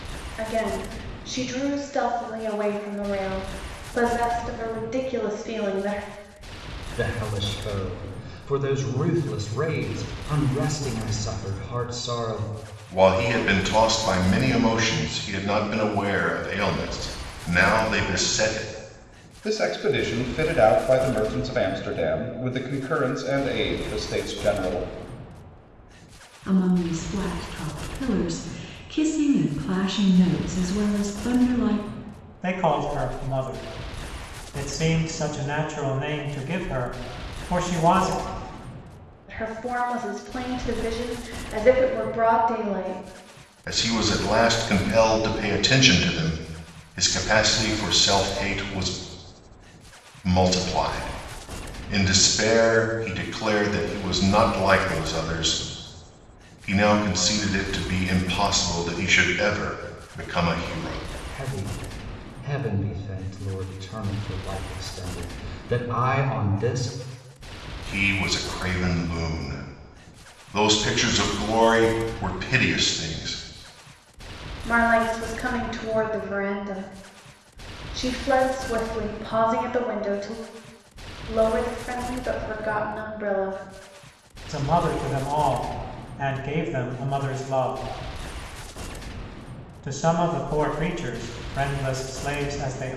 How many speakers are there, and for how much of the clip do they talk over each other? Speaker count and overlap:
six, no overlap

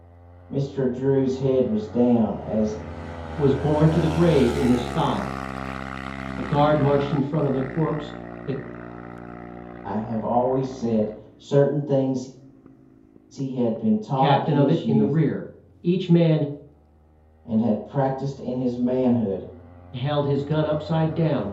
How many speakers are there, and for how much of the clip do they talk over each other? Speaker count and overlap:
two, about 5%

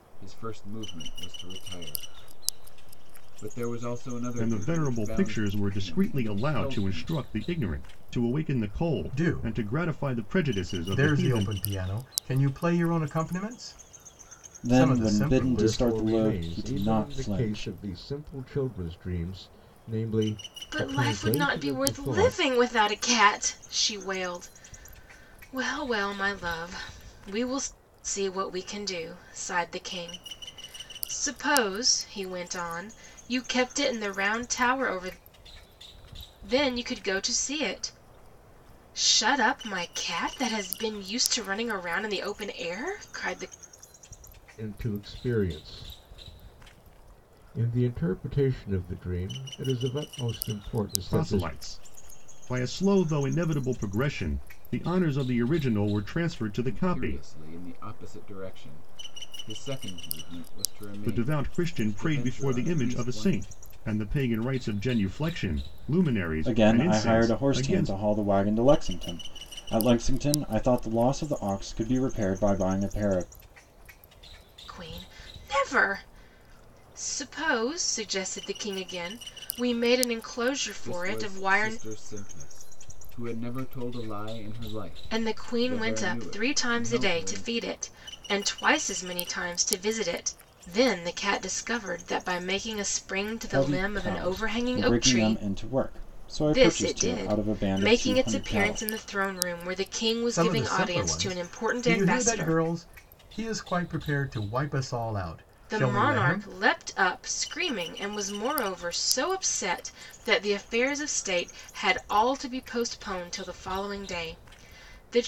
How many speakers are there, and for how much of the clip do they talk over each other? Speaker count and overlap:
six, about 23%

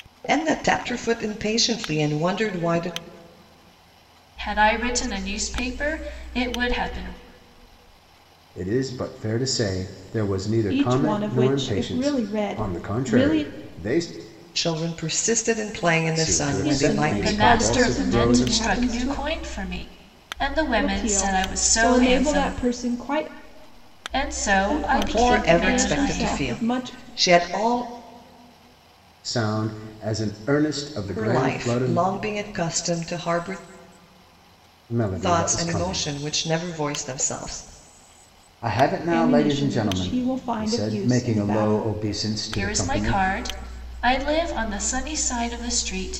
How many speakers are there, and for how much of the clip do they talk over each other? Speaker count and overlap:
four, about 33%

